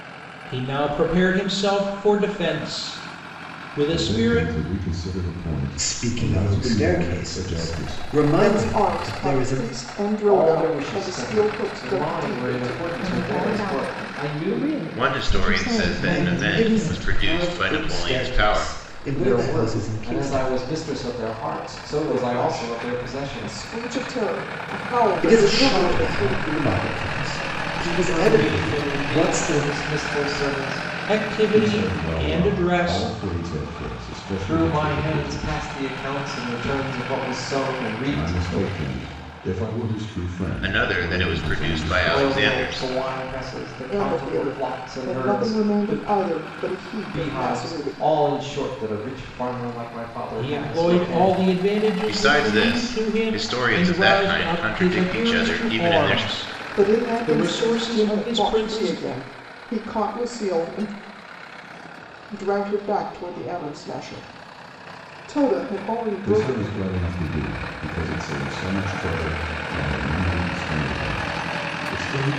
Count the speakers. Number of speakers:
7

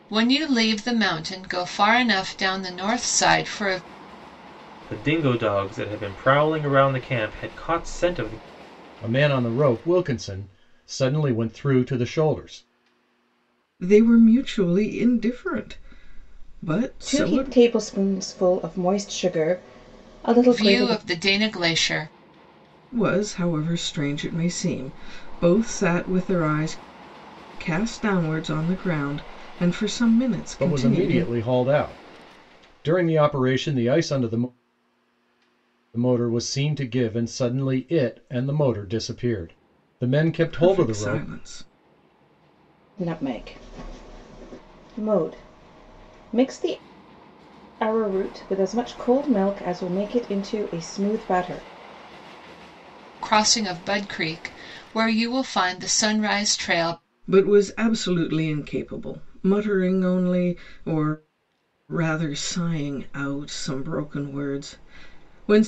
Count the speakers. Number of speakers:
5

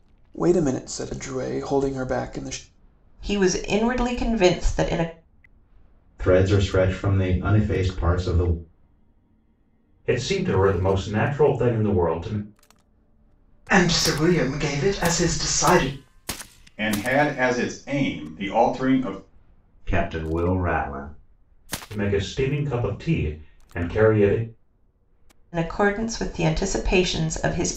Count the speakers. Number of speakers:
7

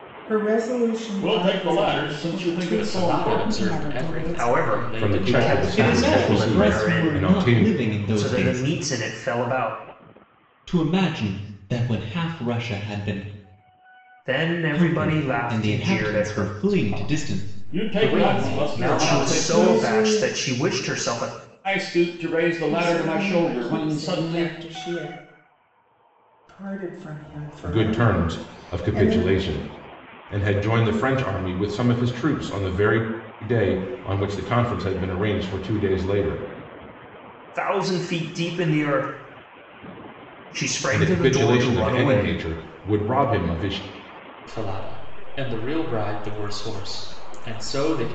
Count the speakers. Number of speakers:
7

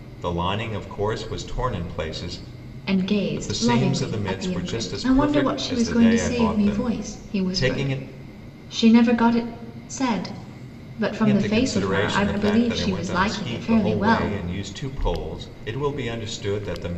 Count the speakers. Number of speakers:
2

